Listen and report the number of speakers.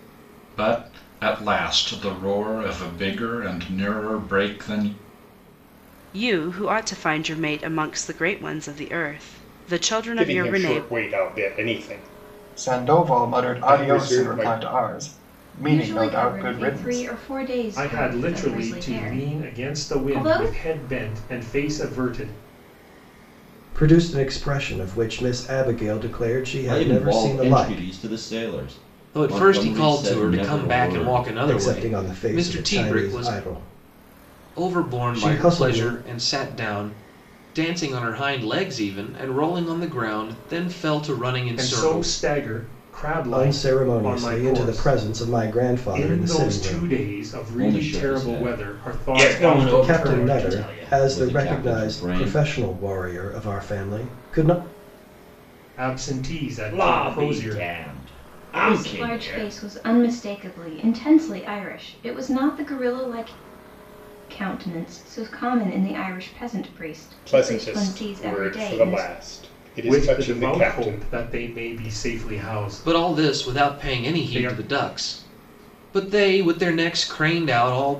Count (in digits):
9